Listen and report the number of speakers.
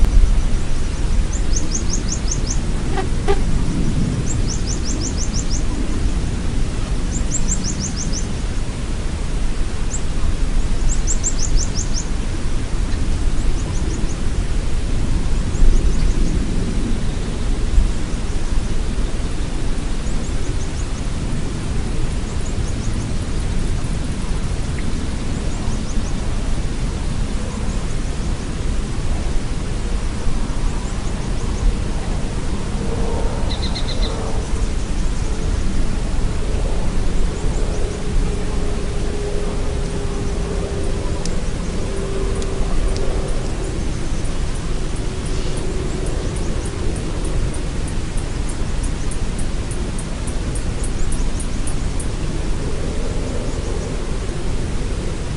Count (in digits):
0